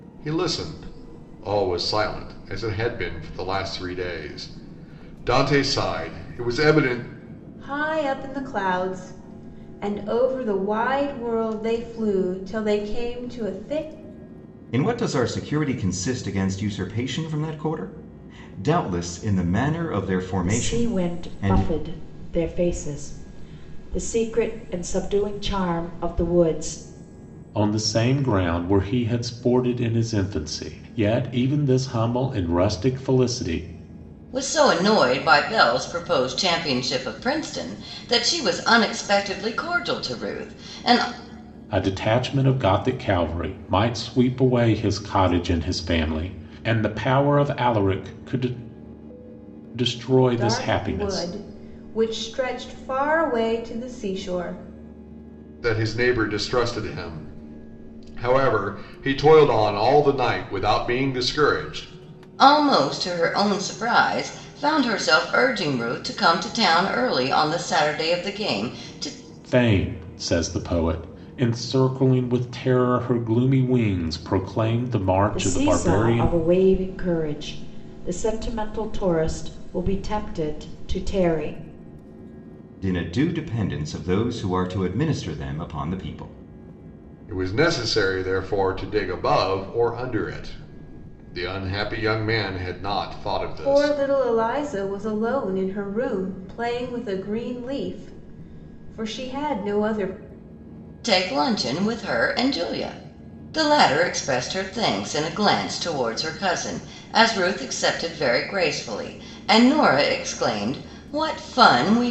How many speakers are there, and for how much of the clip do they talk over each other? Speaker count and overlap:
six, about 3%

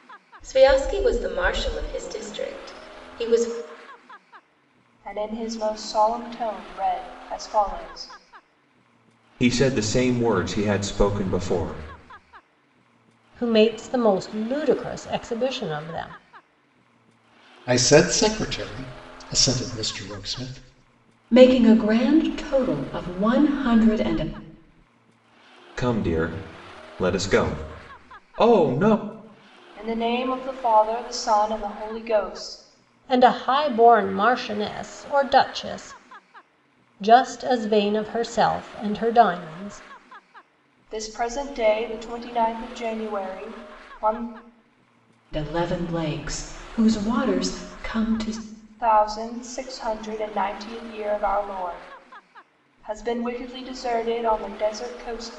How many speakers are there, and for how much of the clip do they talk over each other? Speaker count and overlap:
six, no overlap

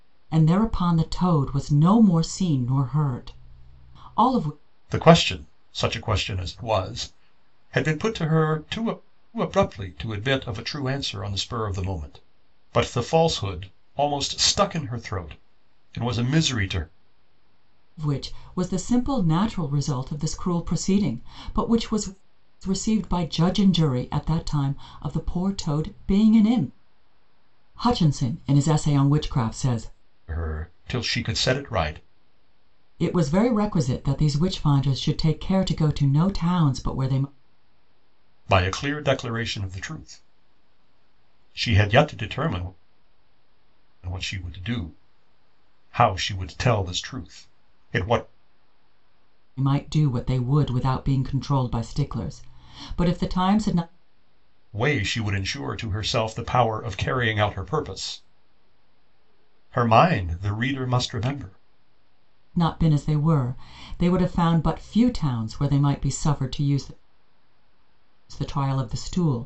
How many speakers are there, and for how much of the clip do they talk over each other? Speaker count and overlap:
two, no overlap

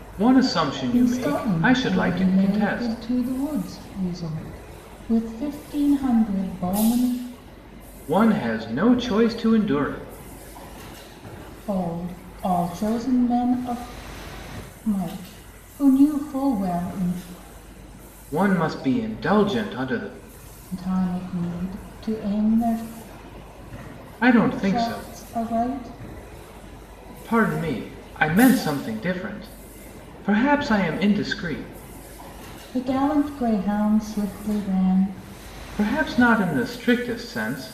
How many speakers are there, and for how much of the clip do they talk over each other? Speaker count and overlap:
two, about 7%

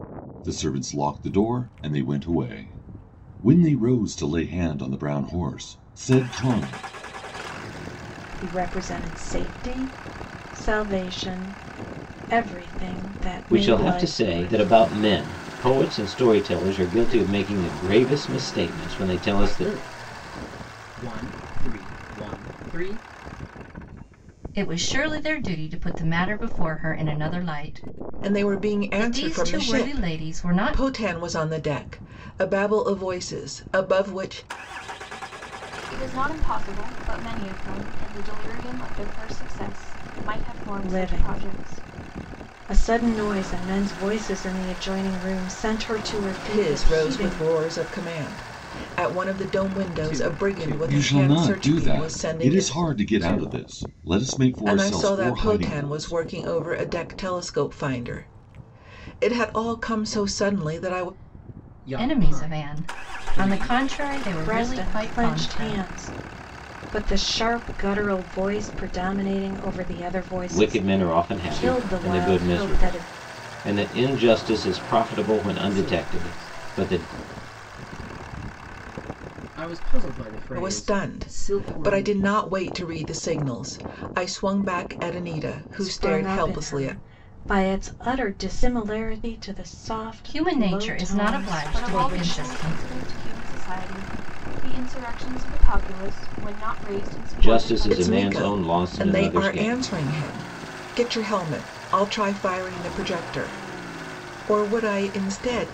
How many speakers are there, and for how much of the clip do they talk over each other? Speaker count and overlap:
seven, about 29%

